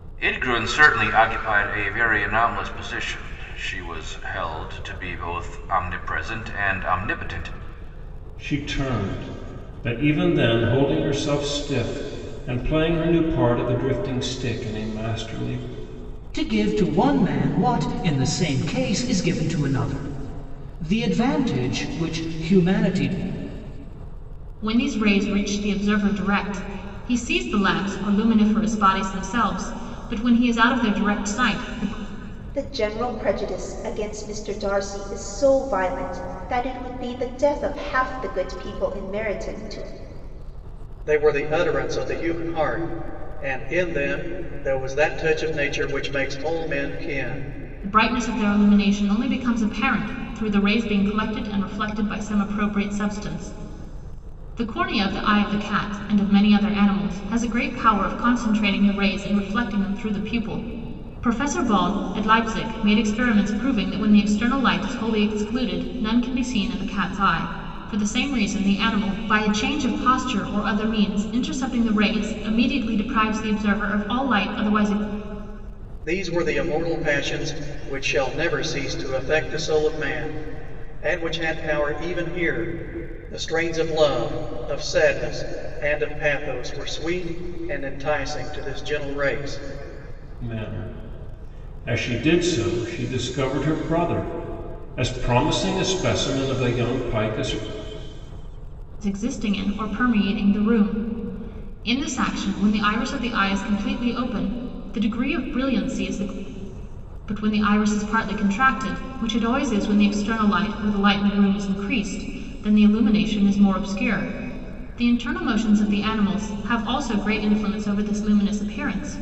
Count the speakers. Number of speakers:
six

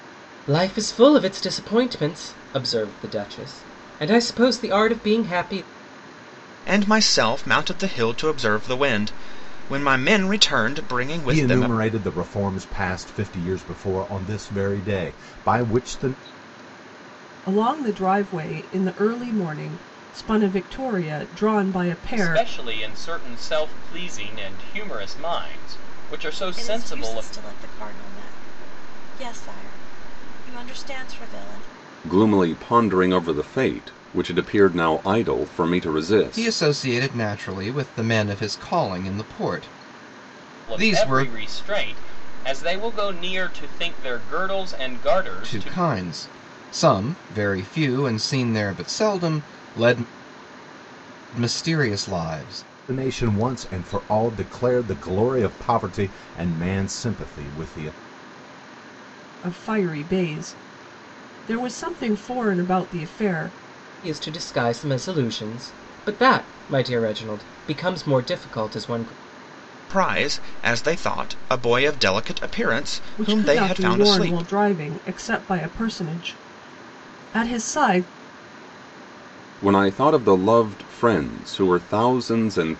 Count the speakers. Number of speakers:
eight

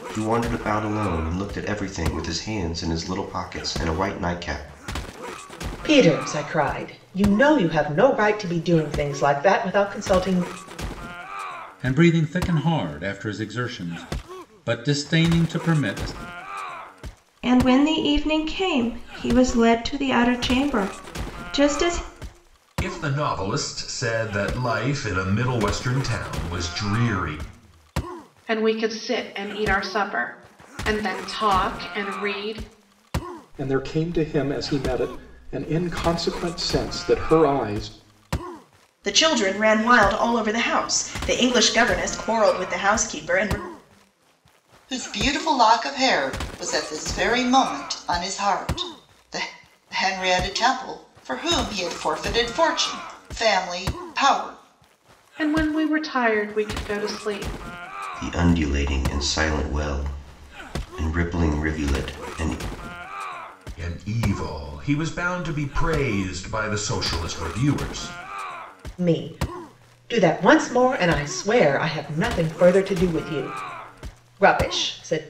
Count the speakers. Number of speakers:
nine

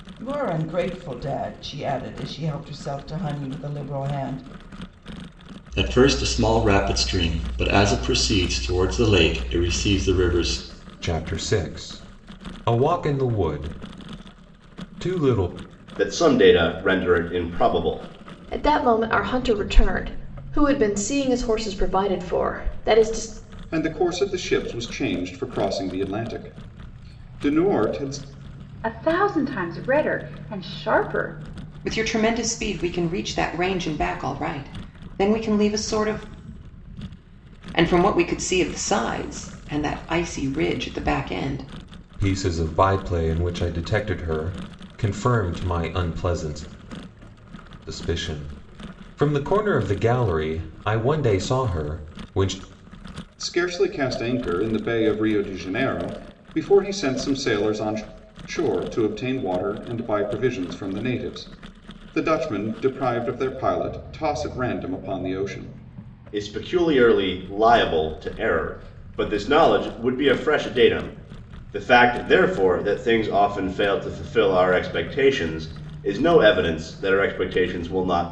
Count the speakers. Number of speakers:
eight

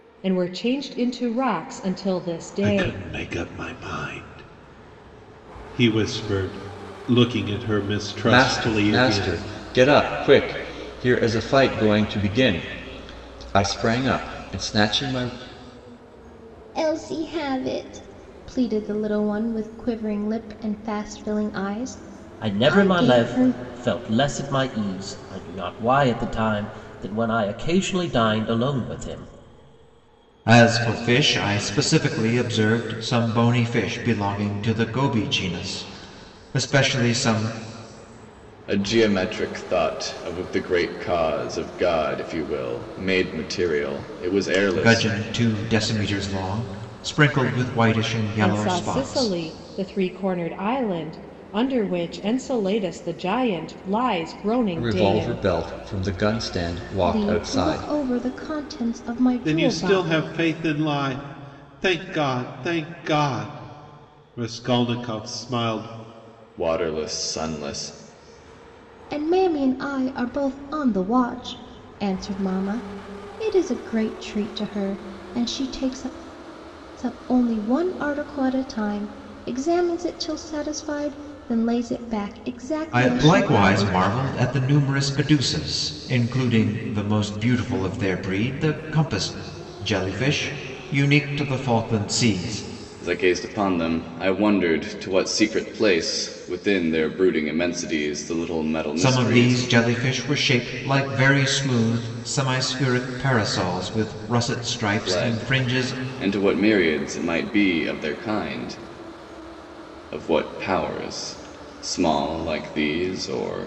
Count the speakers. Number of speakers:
seven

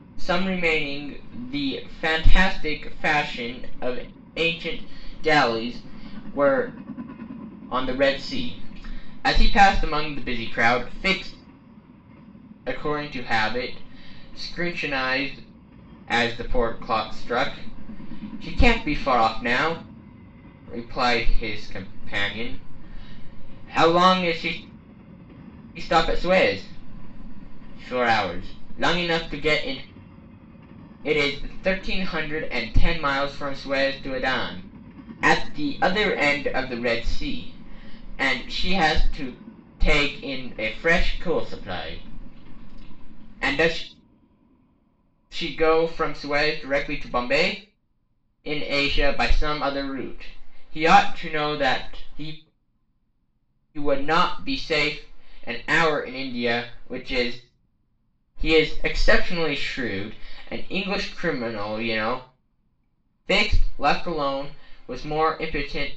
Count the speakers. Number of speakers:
one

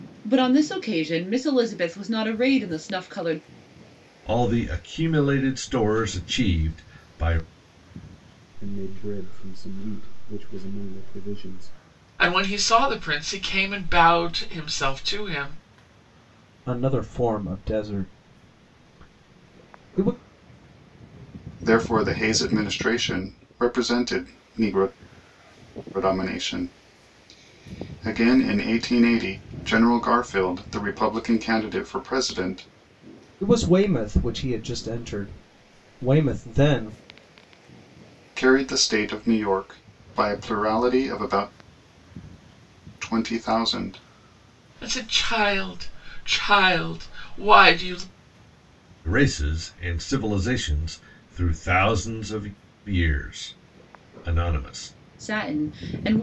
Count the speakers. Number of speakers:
six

